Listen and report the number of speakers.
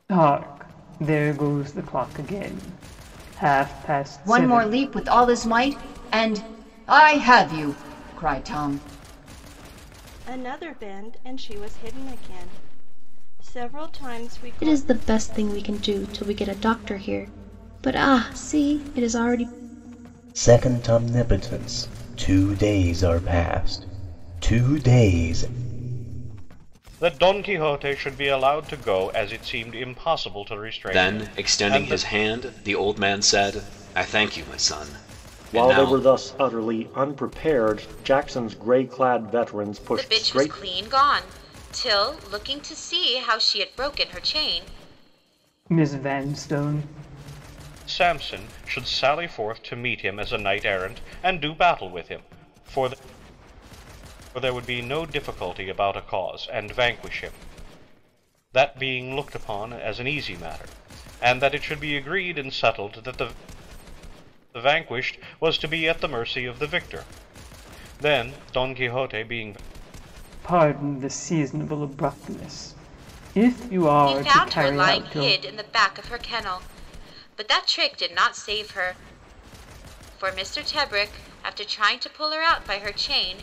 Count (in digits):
9